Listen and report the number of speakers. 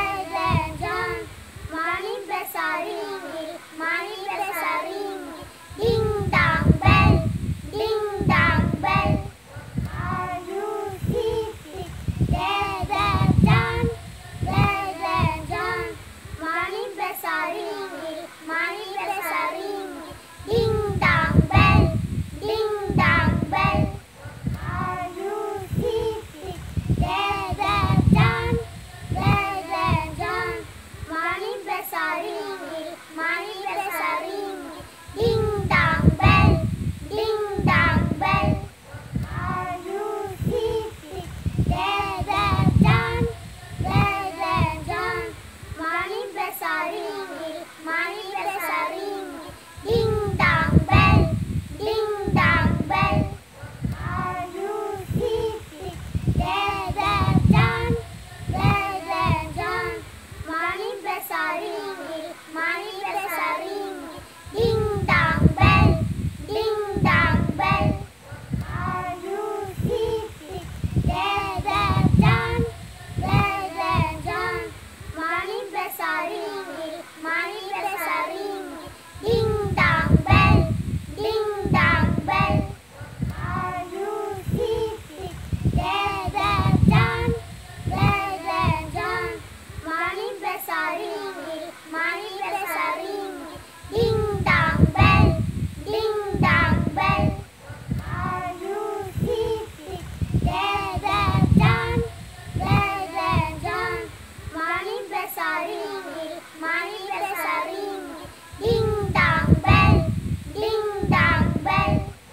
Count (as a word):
zero